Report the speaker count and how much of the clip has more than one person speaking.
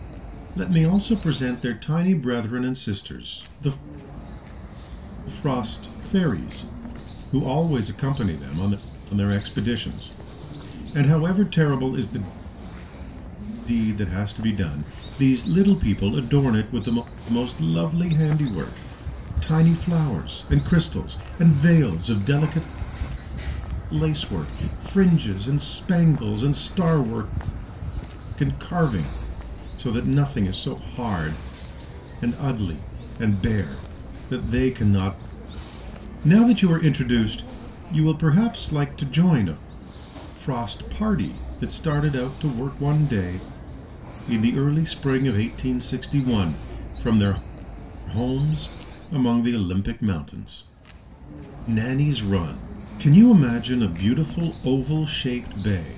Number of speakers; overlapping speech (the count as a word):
one, no overlap